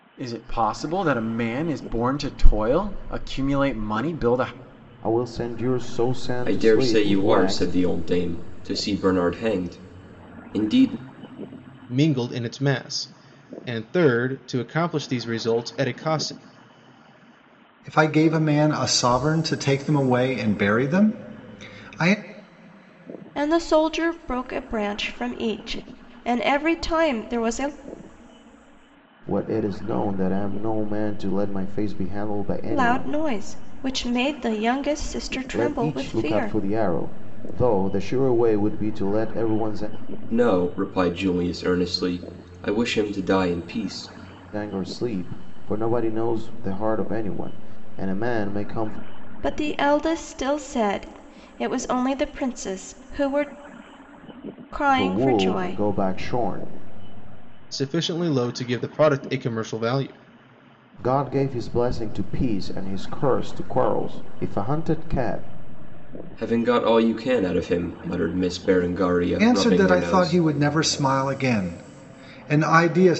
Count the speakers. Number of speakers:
six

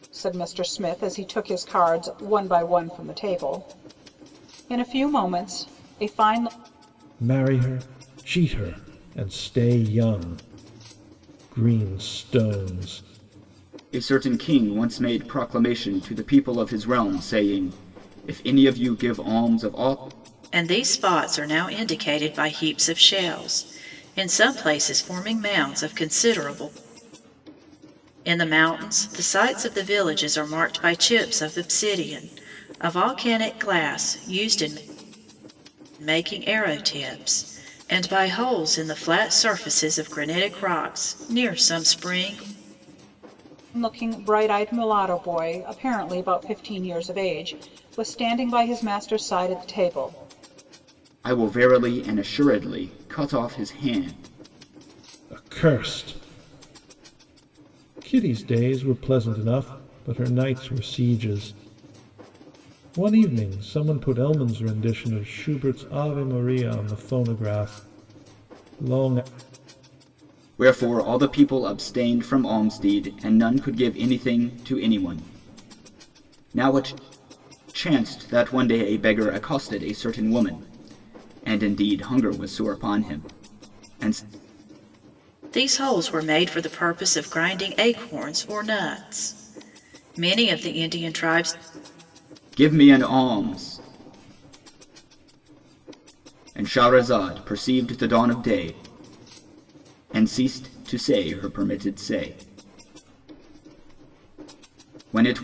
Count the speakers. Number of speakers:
four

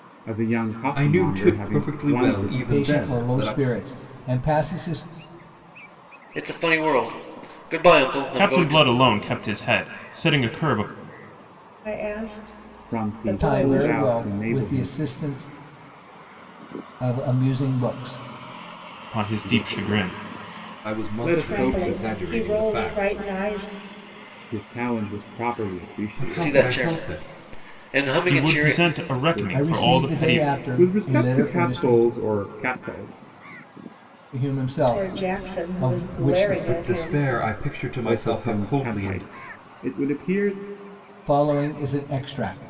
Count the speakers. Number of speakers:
six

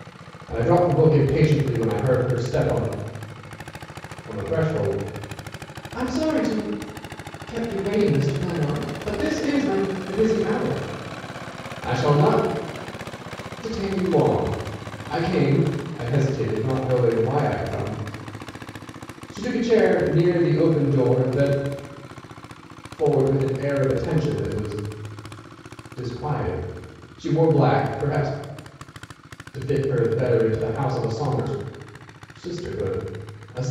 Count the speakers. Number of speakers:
one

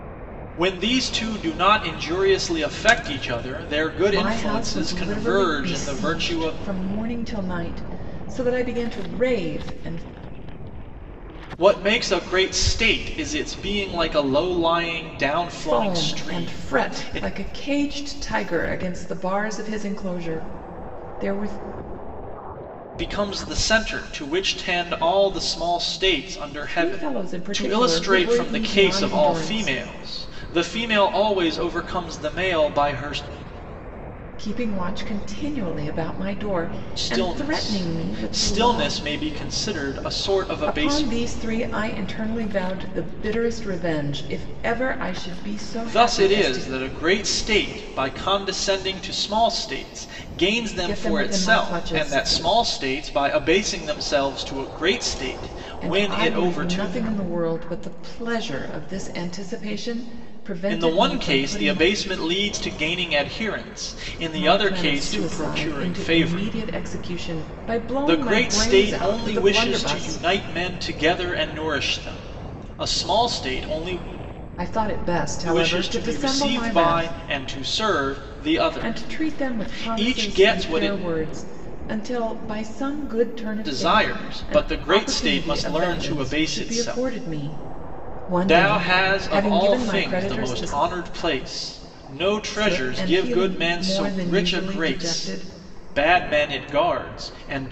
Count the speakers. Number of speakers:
two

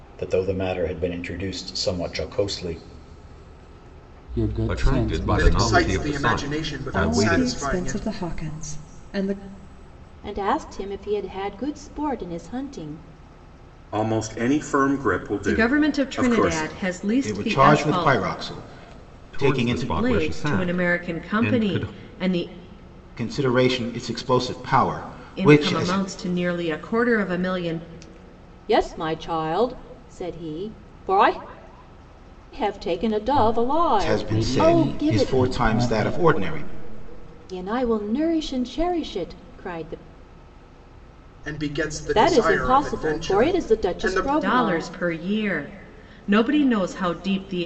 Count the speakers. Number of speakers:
nine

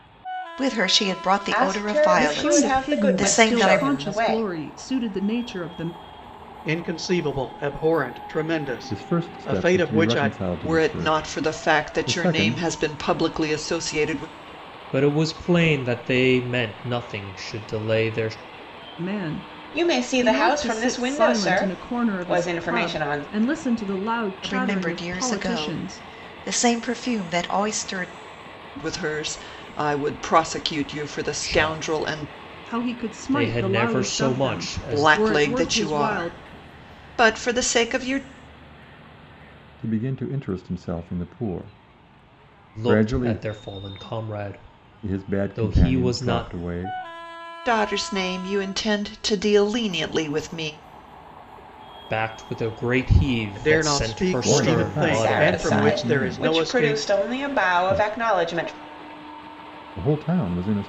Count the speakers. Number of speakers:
seven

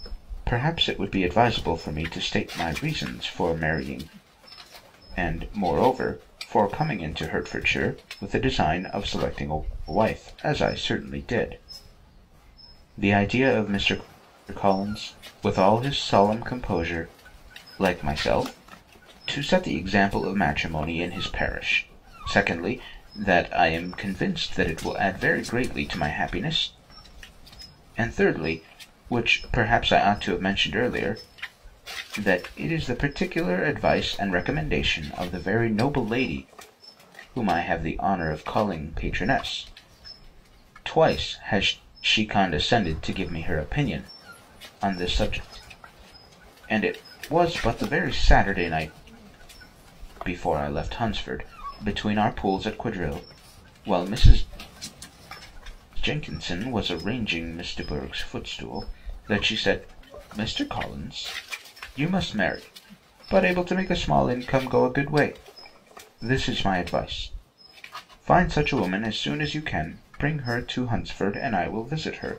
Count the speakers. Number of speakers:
one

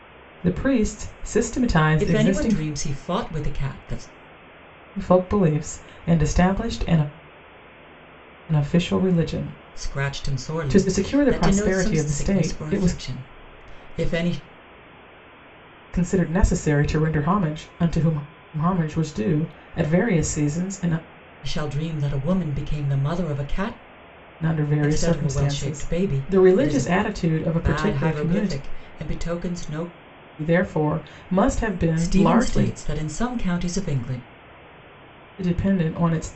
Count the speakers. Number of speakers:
two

